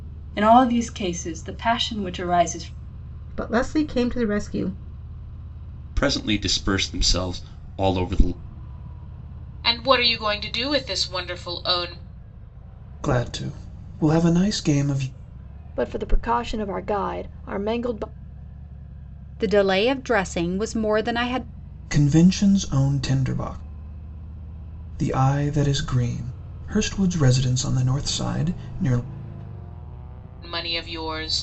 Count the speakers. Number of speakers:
7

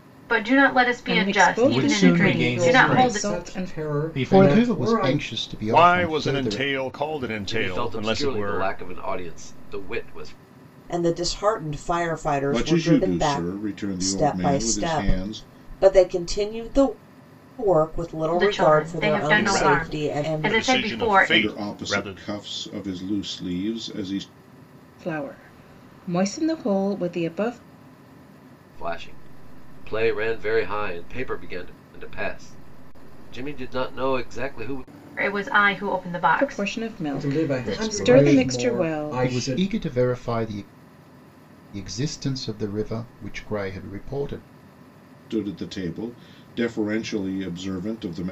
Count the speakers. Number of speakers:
9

